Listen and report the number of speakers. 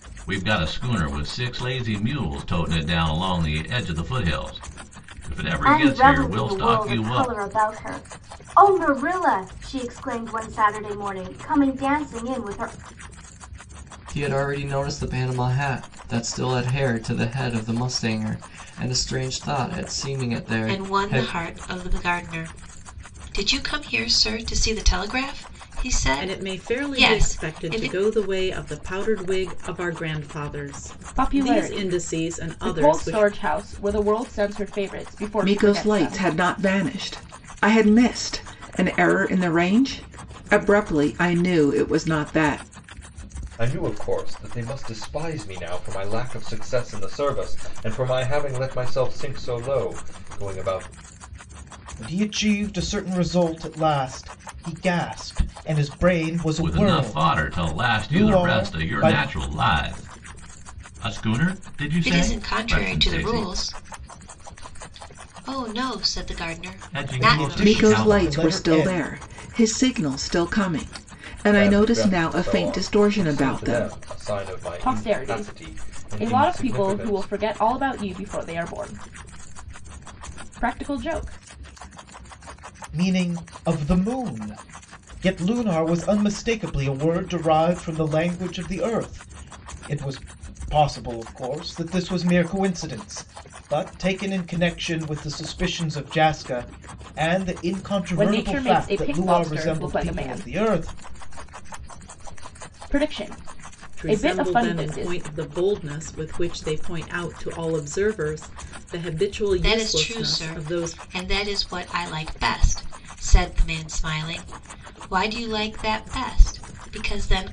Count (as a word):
nine